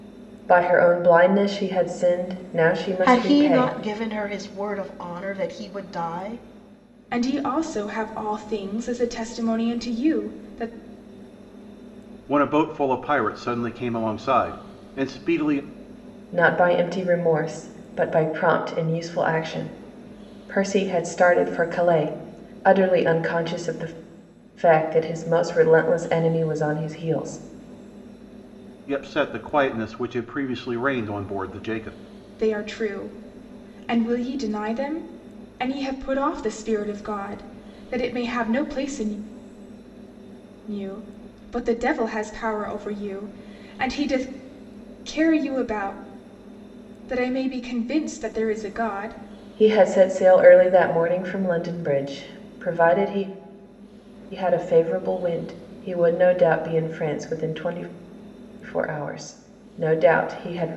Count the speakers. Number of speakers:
four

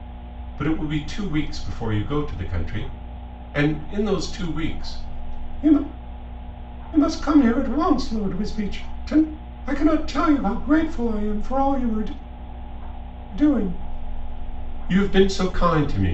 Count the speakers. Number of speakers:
one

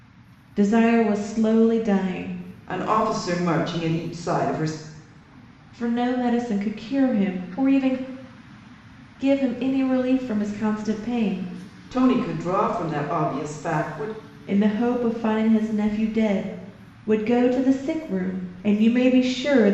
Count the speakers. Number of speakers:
two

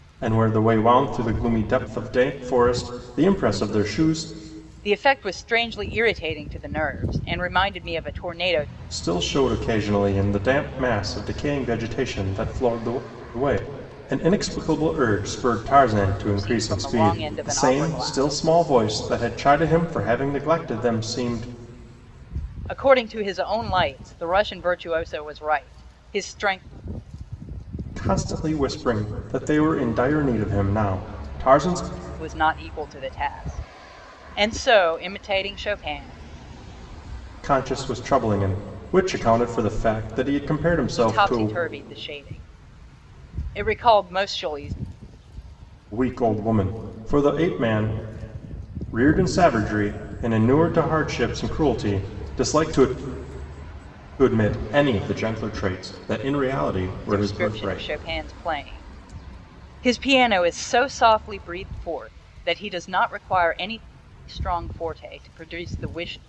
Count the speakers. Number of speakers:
two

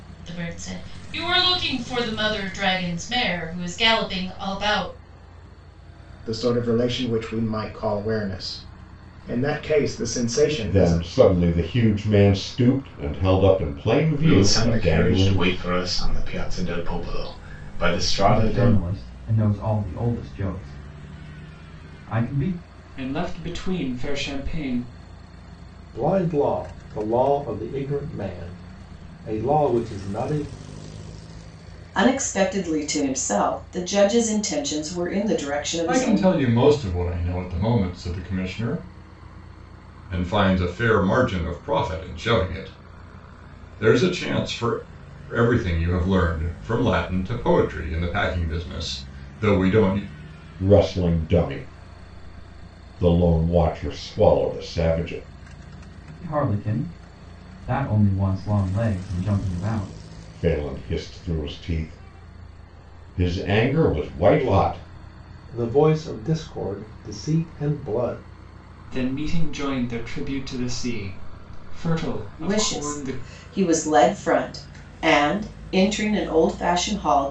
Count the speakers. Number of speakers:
nine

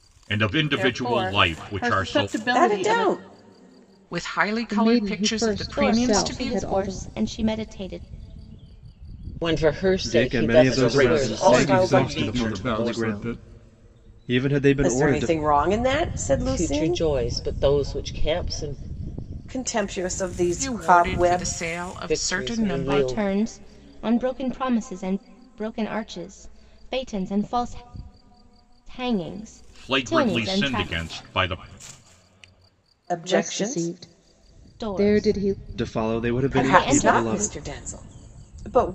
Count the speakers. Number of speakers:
ten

